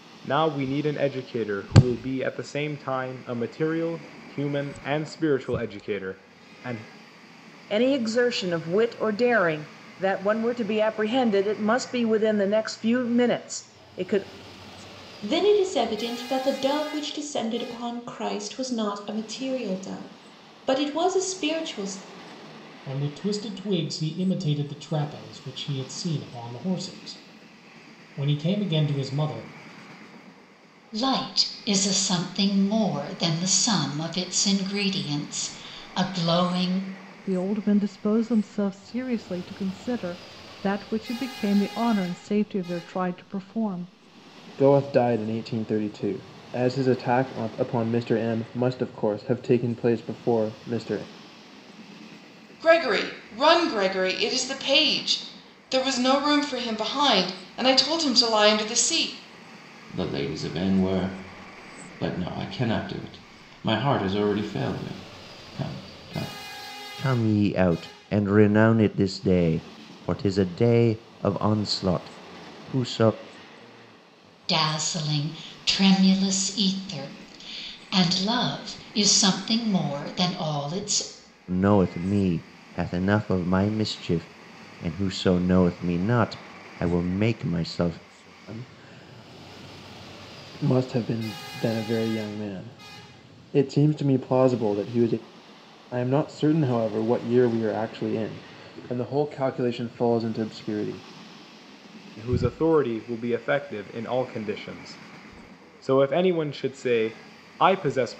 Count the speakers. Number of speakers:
10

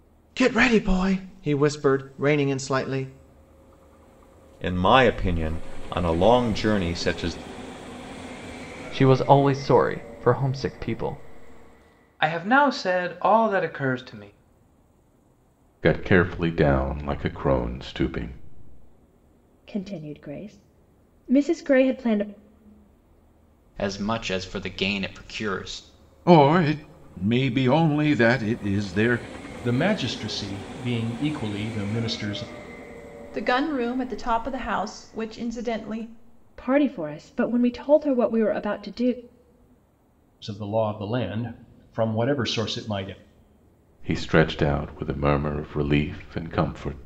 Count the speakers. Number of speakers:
10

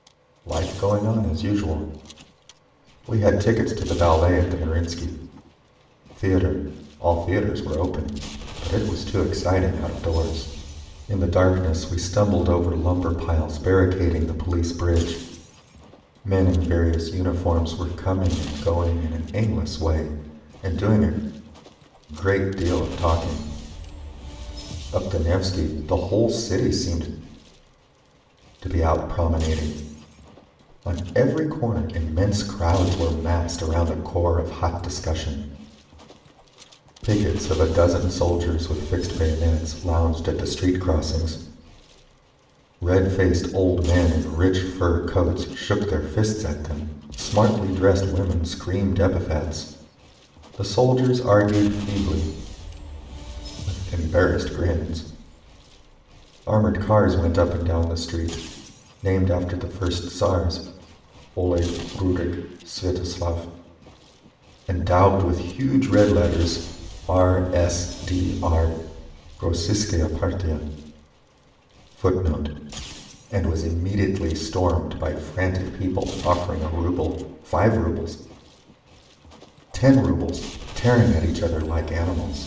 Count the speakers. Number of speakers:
1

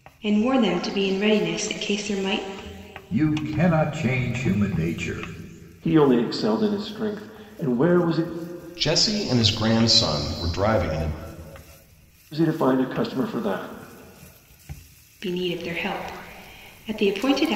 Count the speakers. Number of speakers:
4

